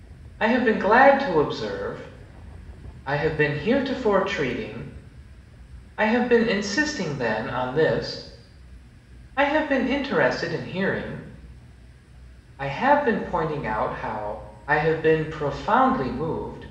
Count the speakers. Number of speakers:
one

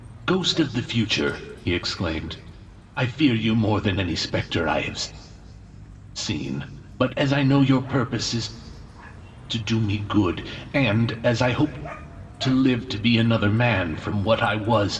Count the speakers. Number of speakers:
one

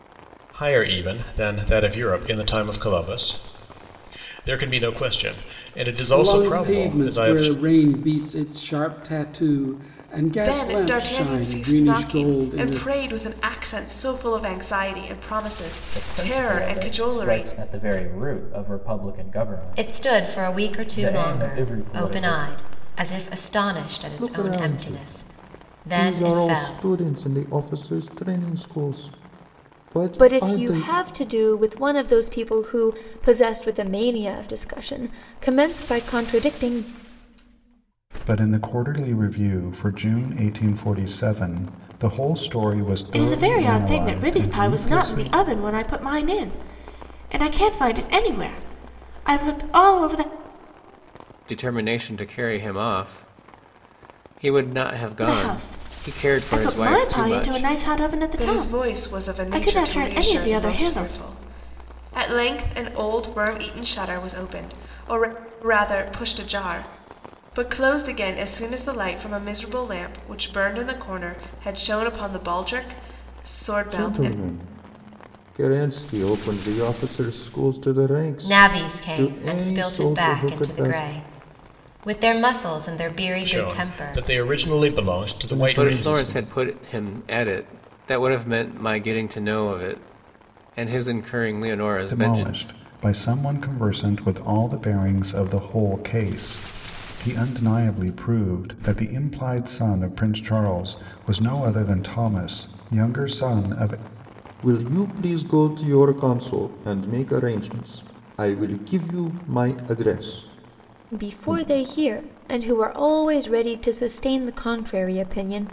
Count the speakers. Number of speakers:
ten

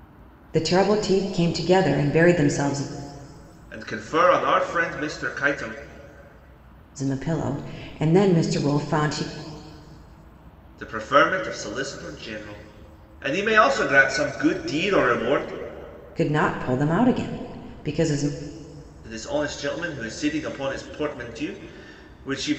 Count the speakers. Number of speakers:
two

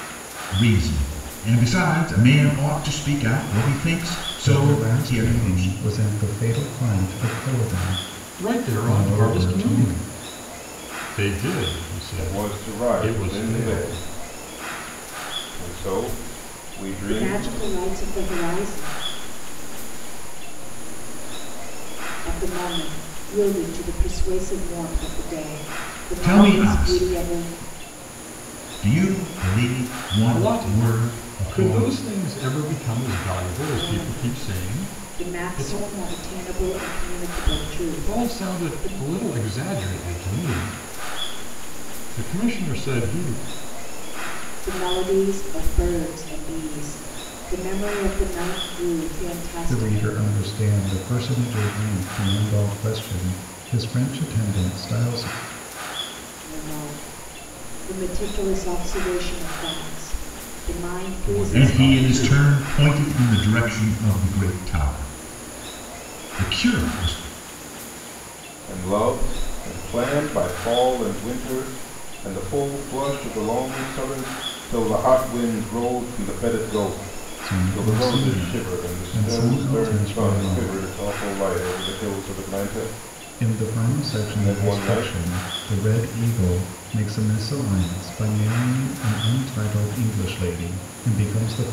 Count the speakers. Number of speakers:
six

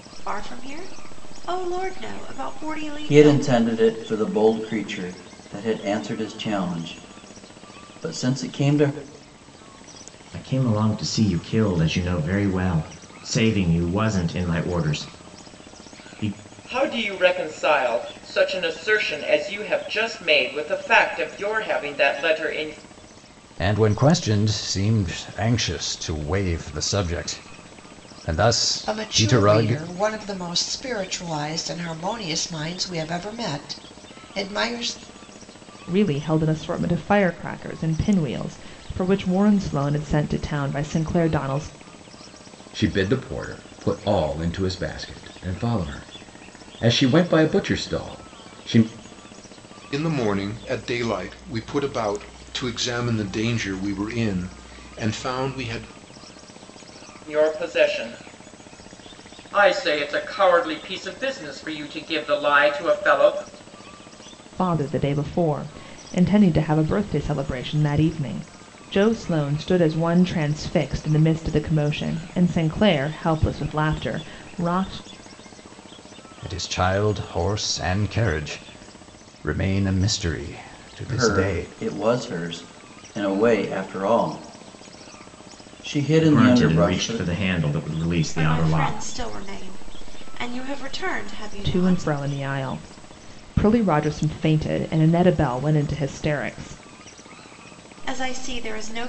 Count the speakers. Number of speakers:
nine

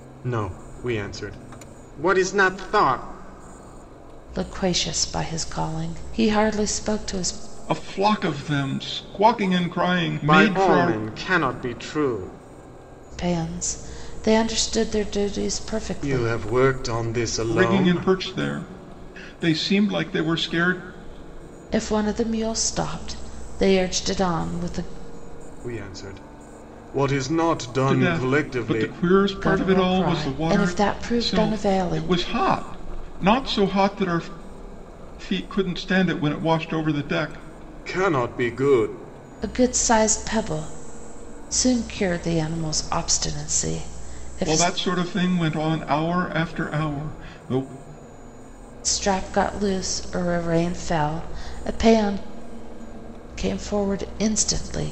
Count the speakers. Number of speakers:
three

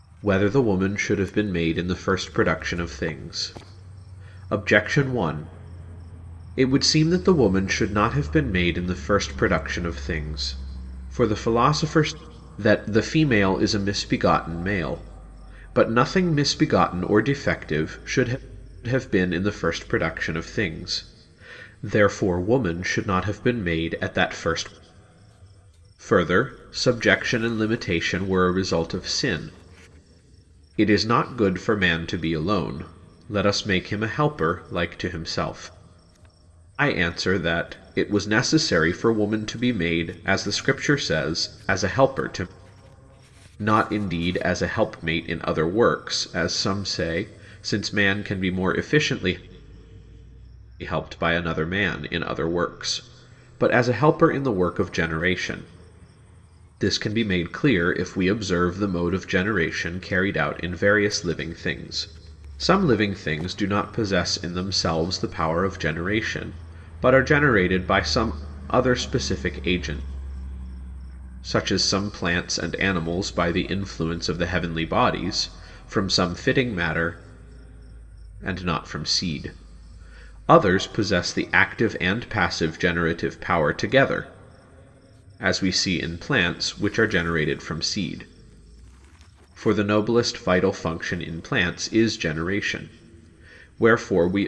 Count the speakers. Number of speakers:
one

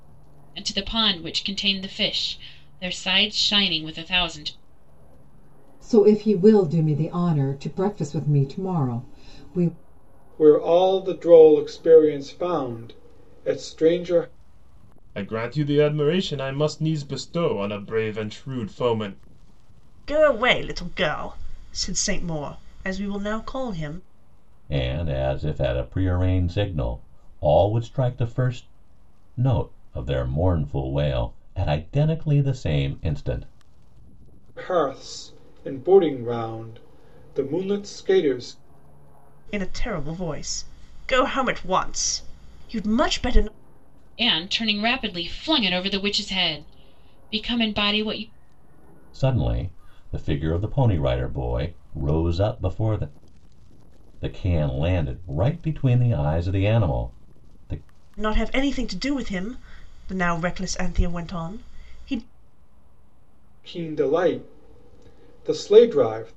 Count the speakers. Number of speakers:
six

